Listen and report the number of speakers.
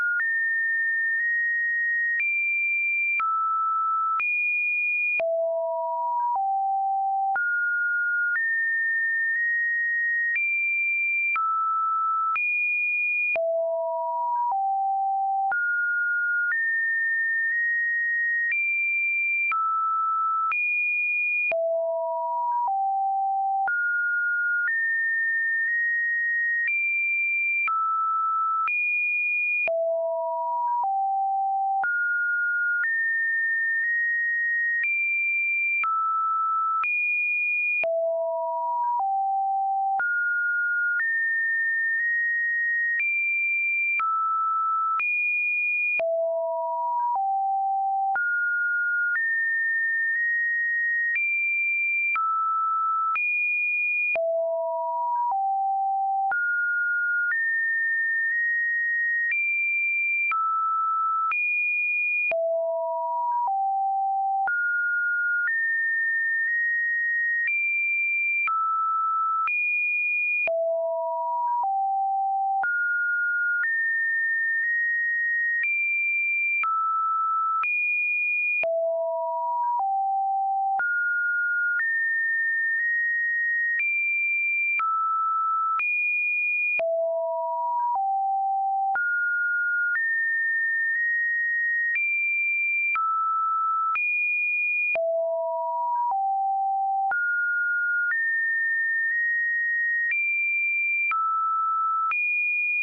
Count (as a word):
zero